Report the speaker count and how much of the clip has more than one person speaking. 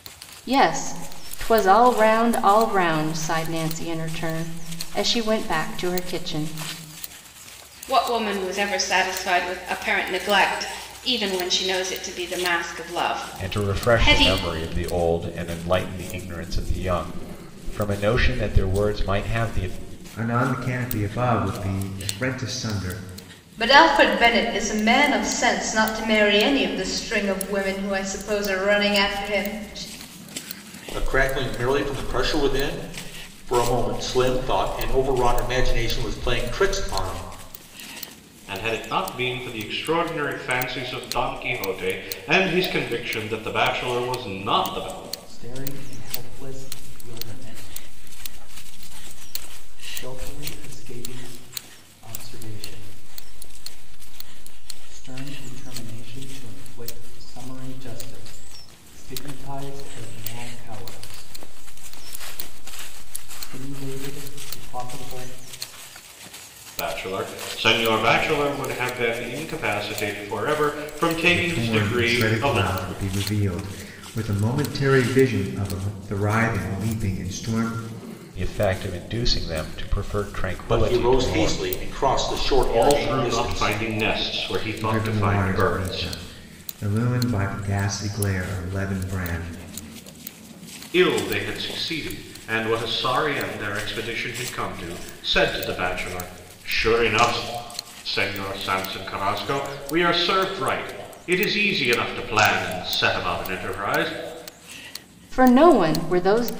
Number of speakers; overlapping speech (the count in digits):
8, about 5%